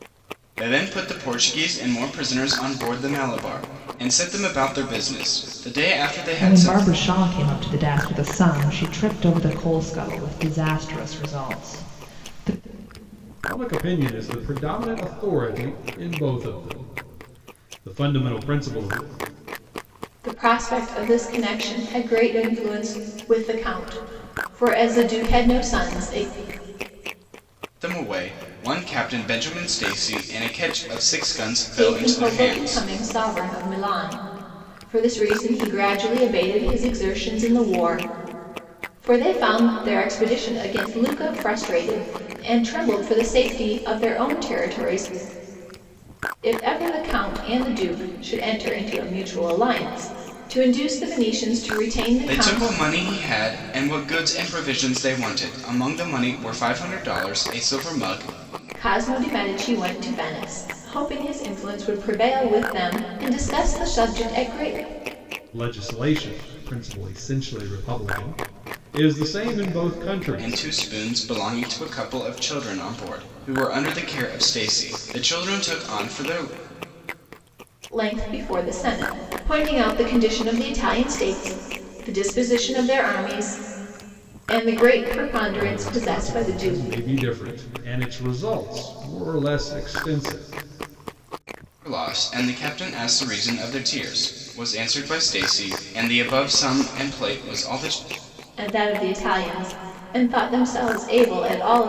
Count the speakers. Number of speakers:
4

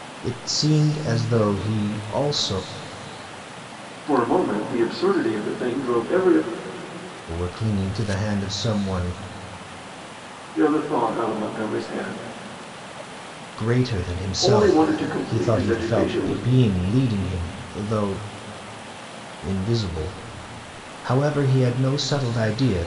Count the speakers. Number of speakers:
2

